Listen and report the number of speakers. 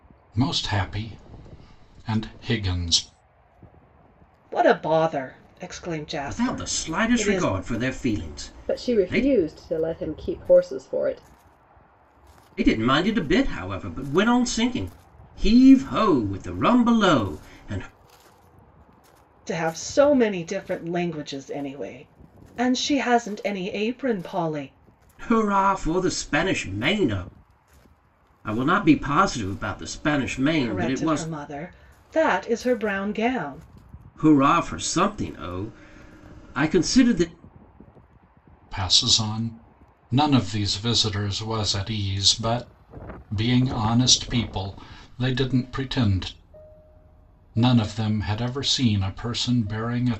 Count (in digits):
4